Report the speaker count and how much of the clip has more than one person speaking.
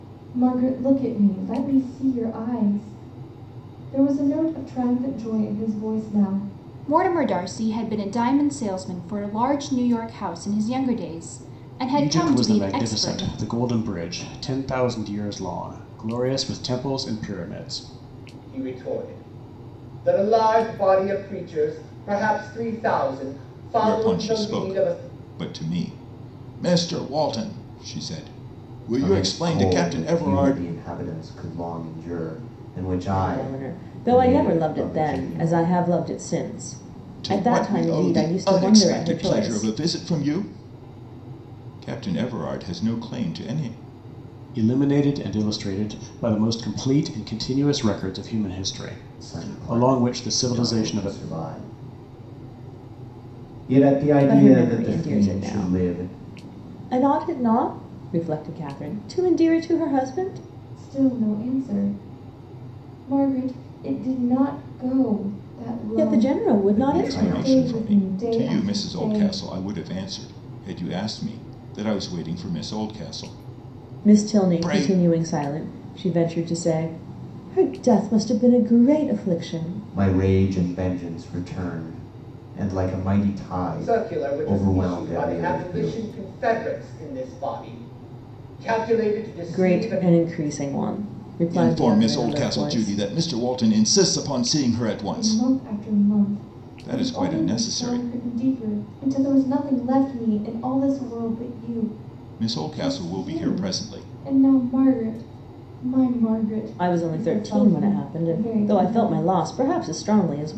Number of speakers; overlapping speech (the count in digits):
7, about 27%